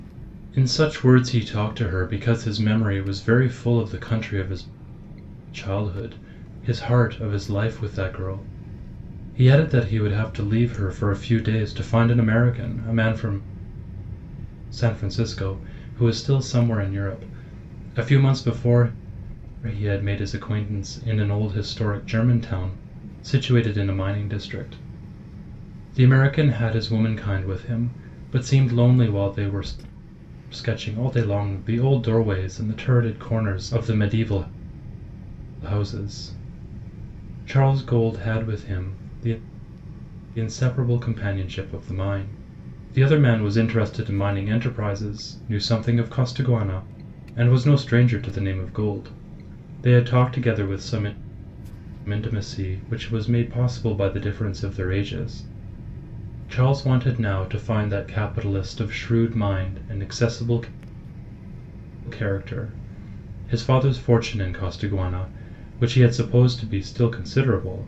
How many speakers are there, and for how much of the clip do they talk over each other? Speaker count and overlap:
one, no overlap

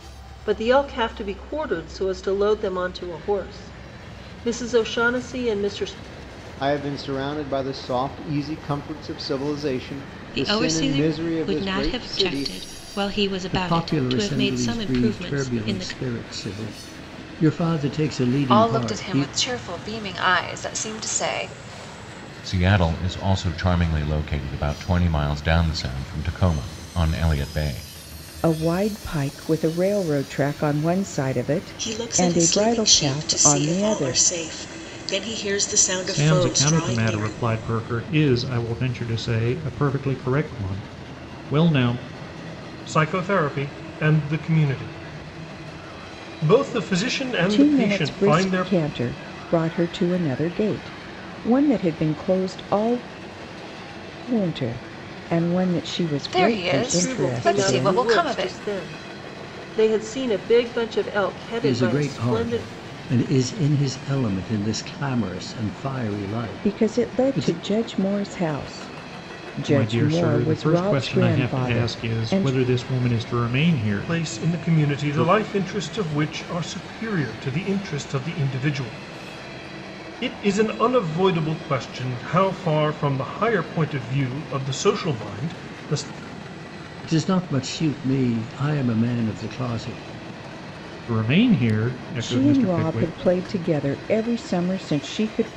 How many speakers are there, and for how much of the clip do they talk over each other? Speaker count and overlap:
ten, about 21%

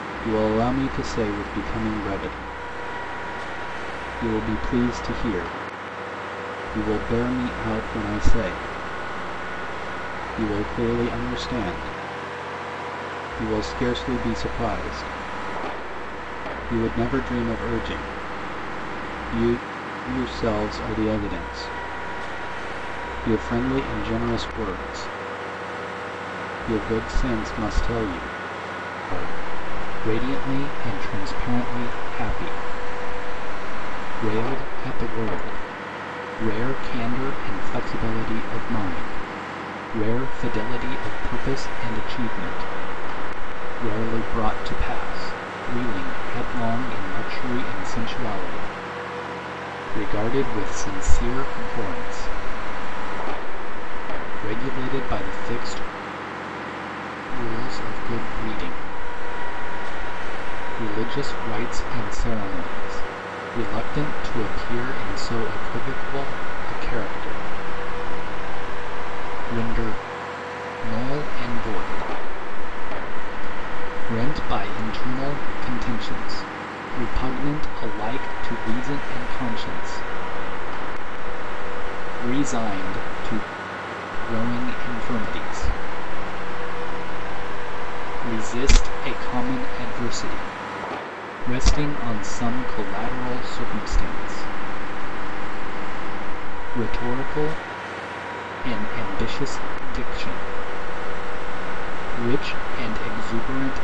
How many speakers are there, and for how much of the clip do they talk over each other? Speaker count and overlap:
one, no overlap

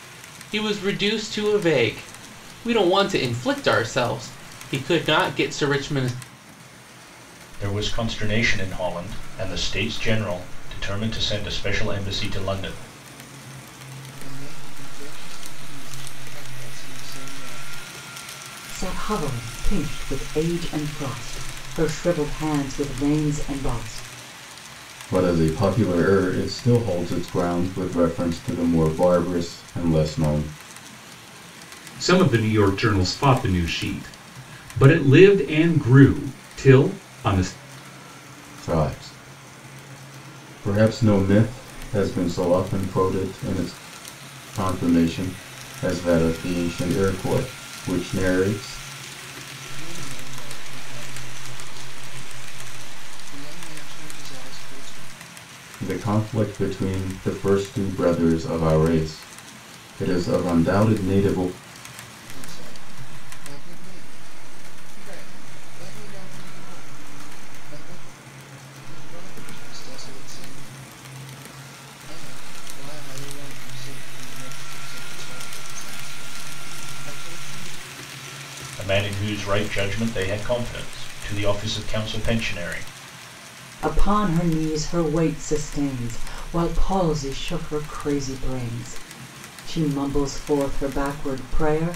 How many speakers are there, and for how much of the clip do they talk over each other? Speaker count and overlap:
six, no overlap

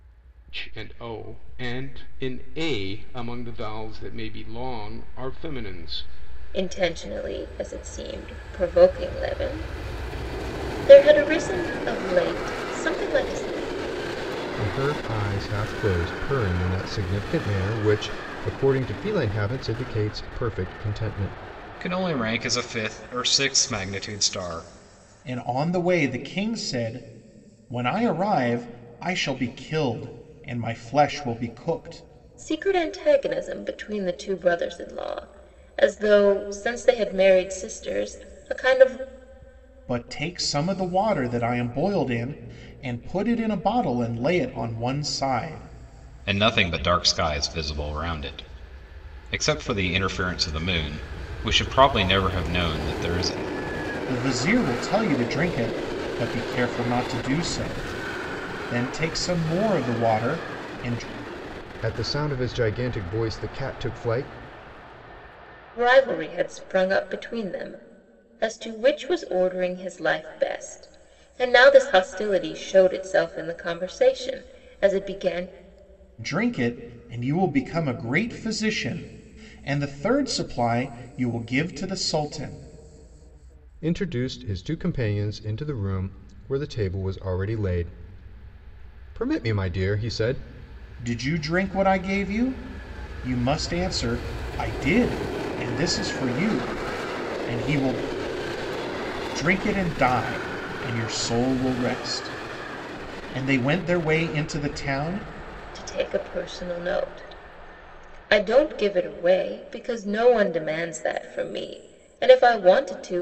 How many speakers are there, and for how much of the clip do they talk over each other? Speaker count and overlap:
five, no overlap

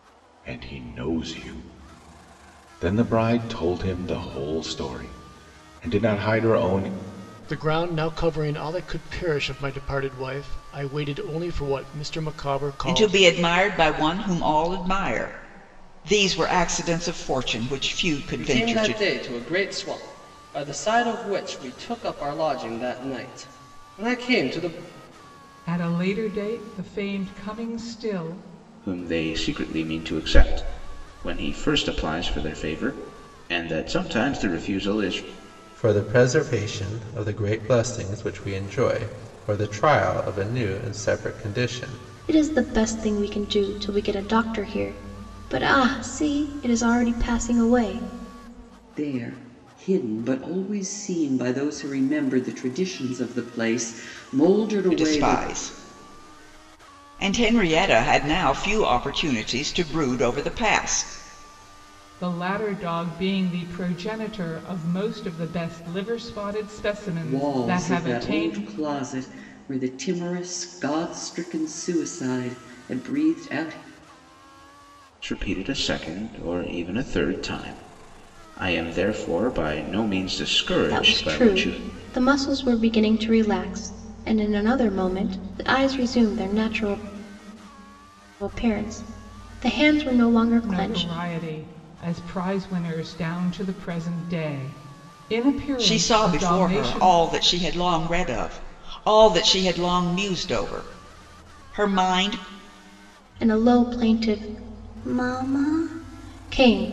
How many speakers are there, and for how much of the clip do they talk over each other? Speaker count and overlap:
nine, about 6%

